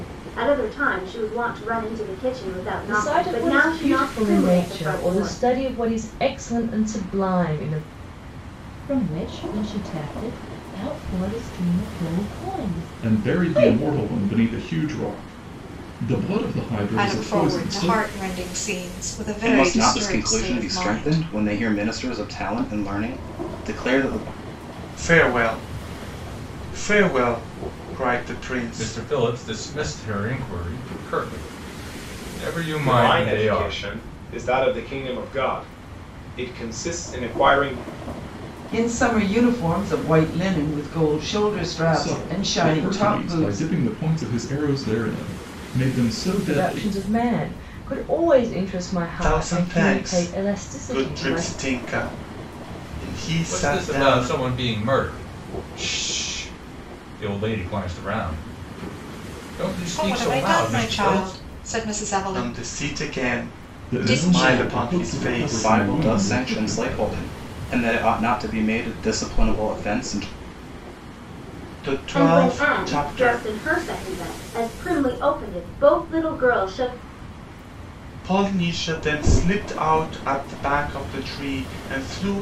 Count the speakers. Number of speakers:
10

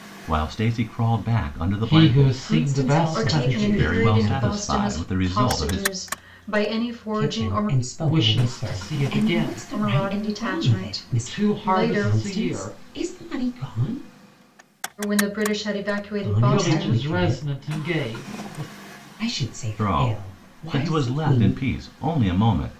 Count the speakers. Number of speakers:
4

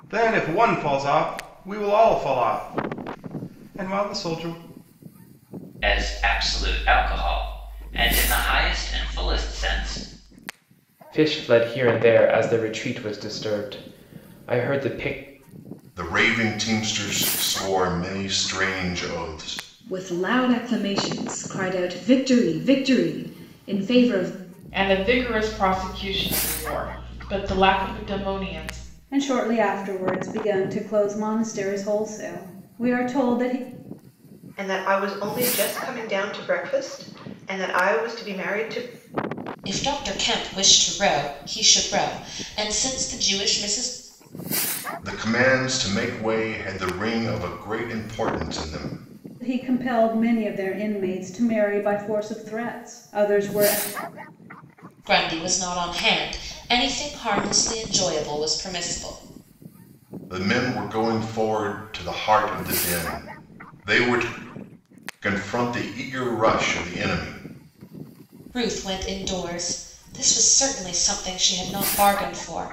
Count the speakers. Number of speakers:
9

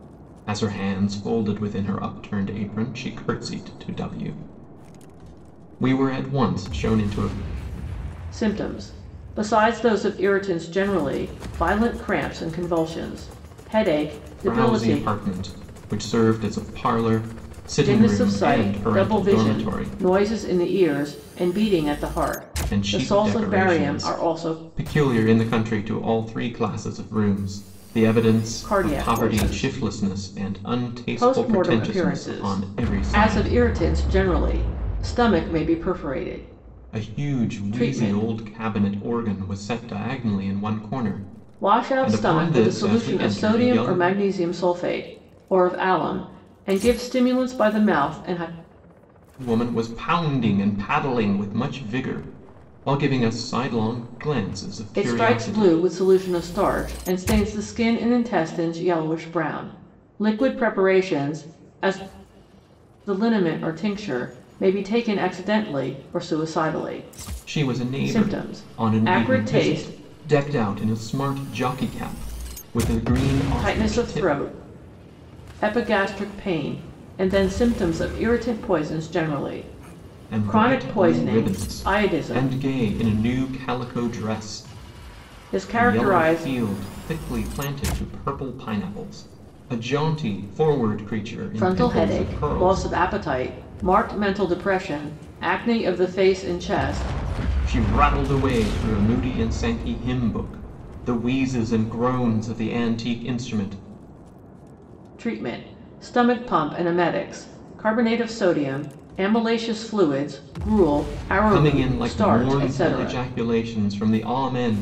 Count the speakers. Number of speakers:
2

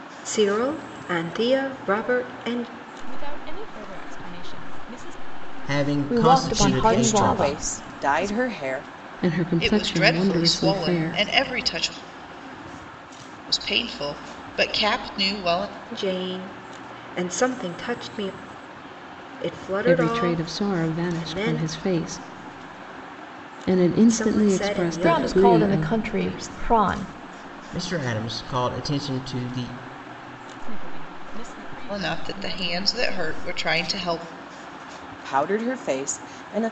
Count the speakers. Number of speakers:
7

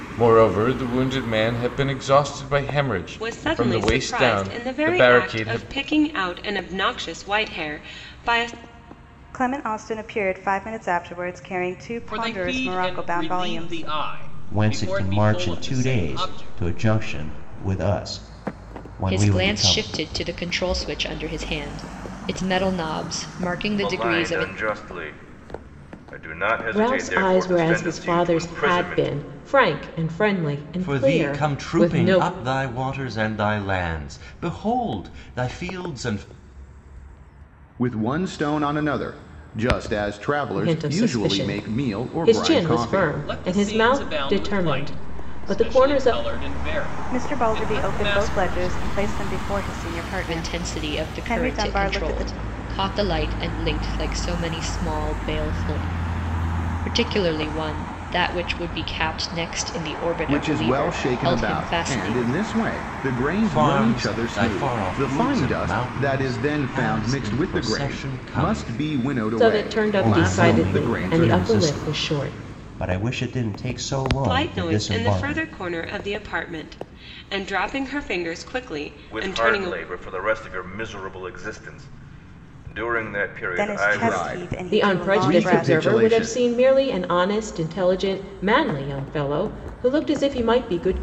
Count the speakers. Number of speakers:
10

